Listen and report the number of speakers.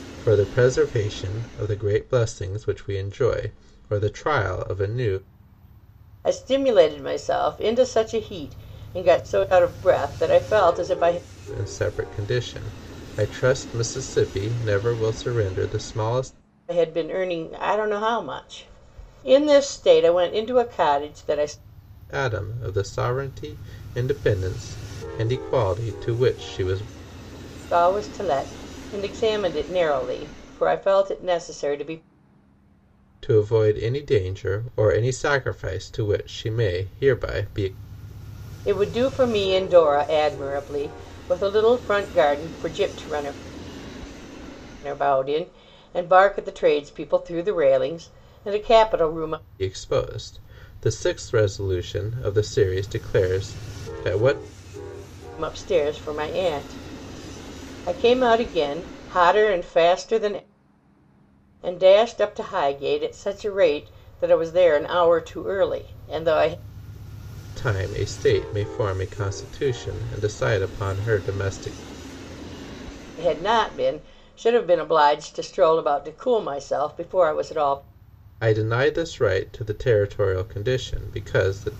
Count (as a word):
two